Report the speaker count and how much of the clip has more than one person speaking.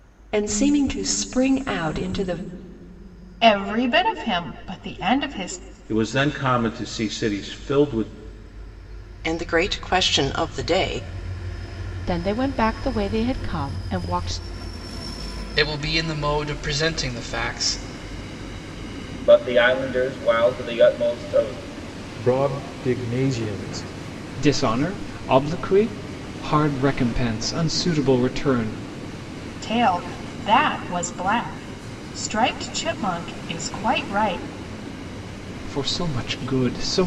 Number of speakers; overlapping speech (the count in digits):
9, no overlap